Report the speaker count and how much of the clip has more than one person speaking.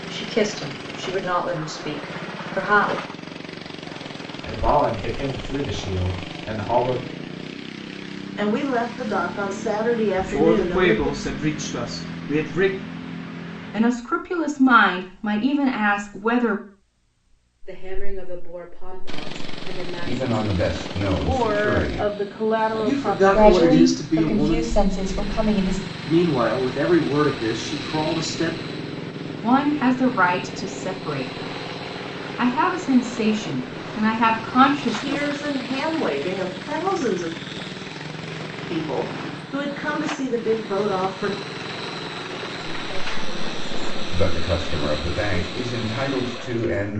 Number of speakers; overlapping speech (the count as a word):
ten, about 13%